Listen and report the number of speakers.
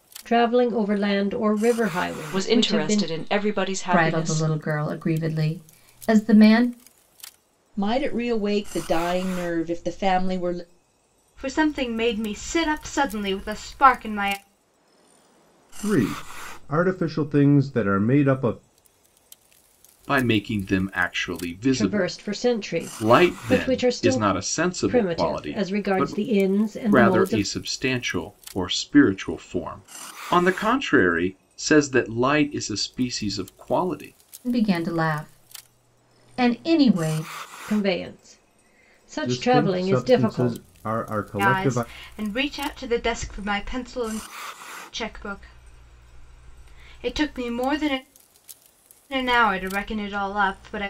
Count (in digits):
7